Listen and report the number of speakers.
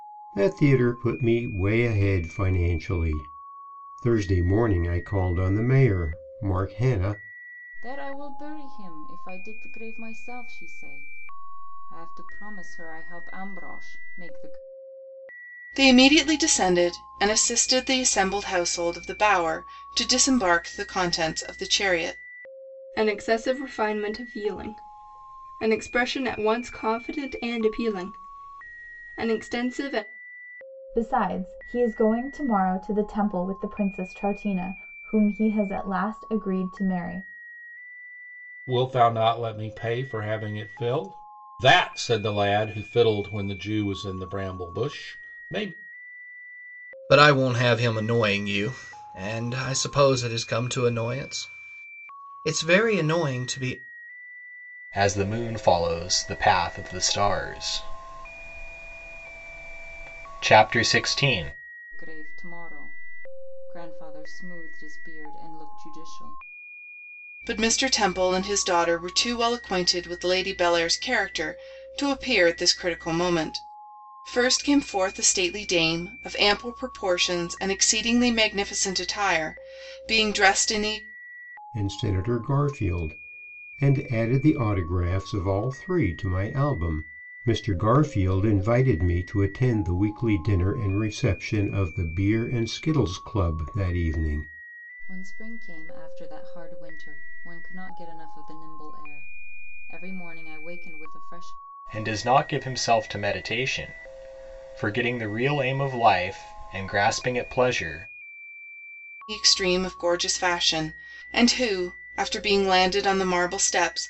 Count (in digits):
8